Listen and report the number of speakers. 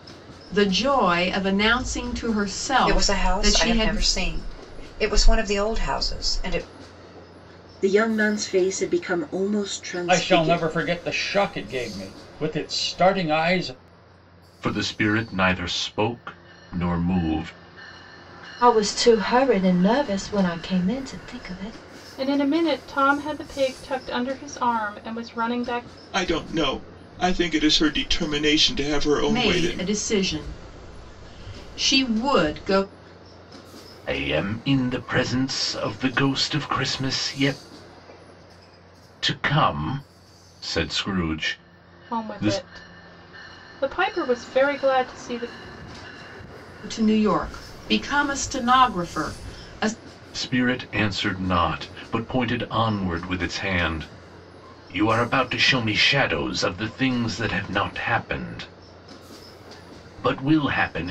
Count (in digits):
8